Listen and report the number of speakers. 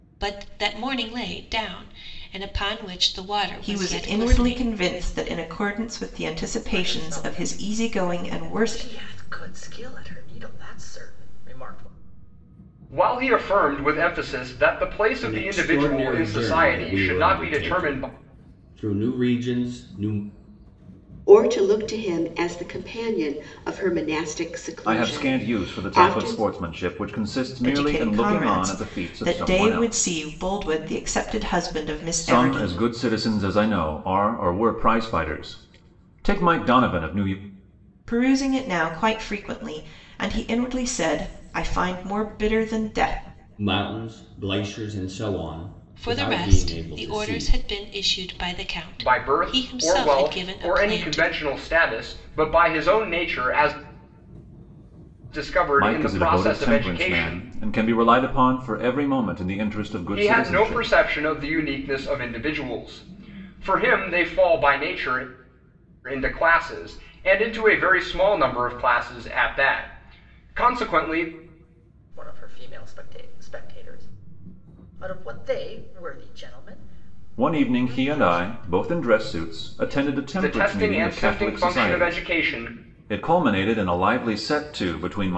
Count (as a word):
seven